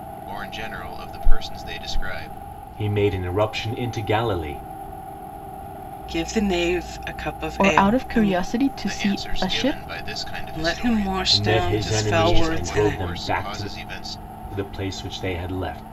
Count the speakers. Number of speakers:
4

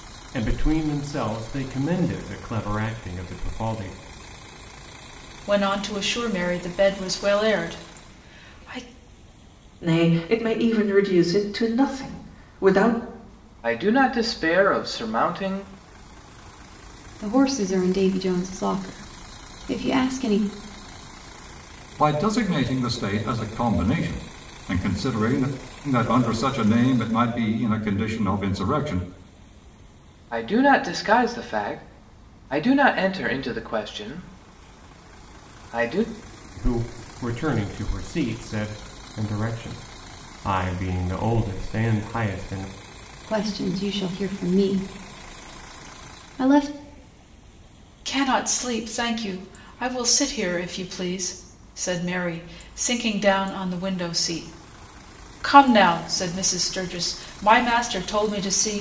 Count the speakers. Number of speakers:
6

